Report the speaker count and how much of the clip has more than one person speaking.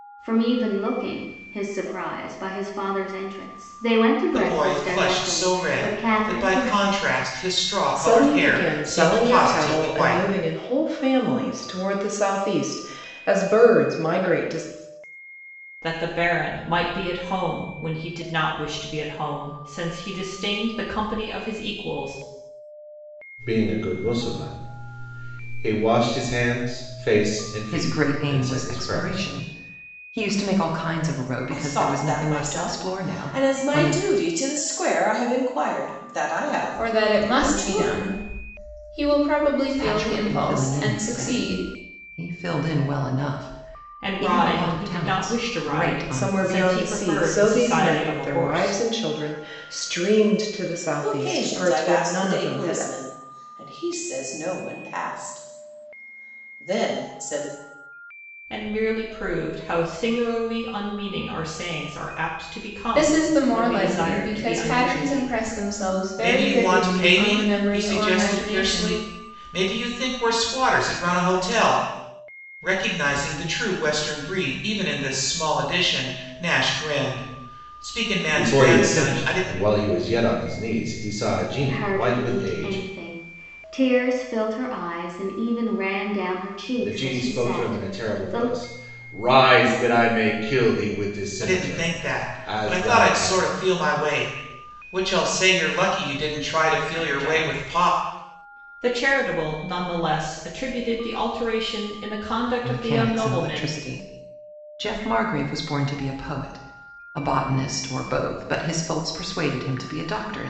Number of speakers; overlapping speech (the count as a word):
eight, about 29%